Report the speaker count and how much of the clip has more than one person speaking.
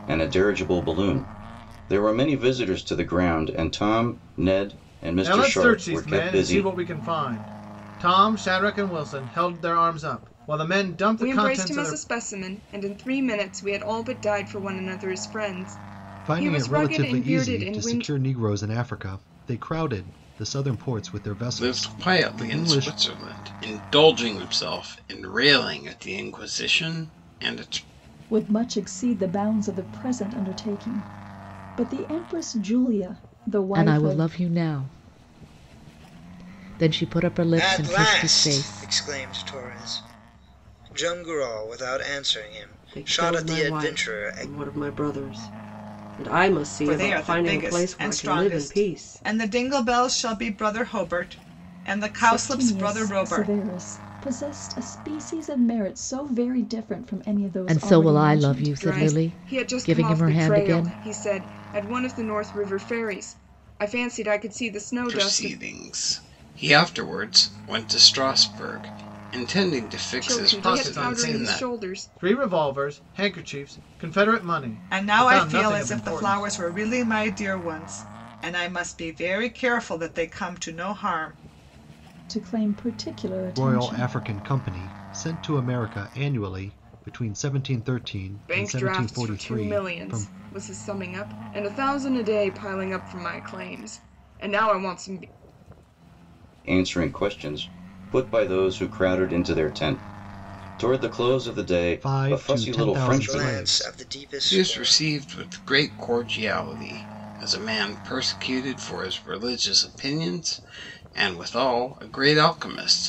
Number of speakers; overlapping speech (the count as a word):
ten, about 23%